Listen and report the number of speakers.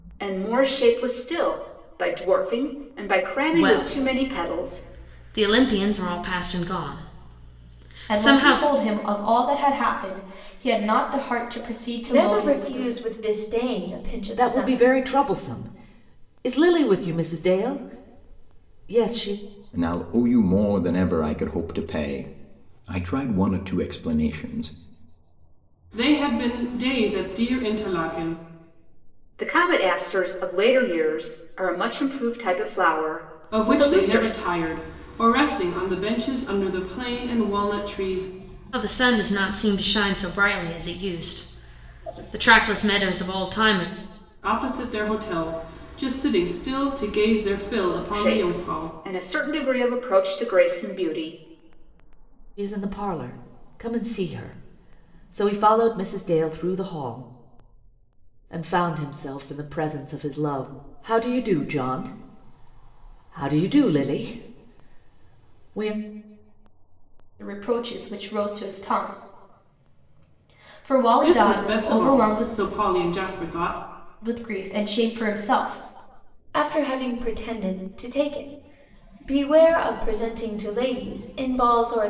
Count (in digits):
7